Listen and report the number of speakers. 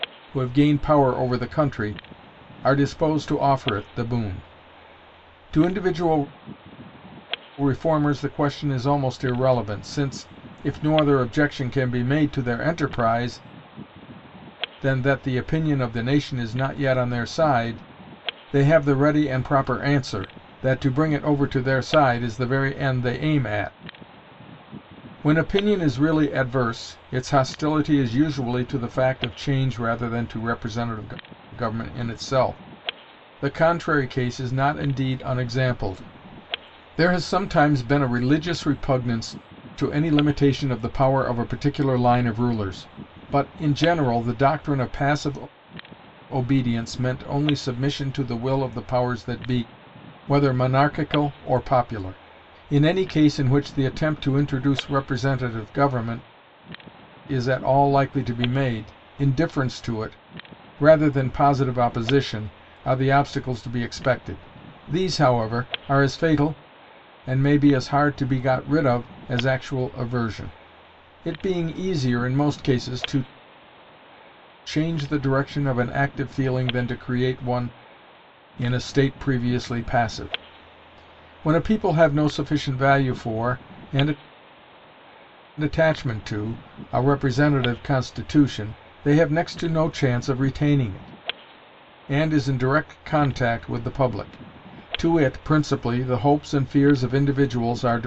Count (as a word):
one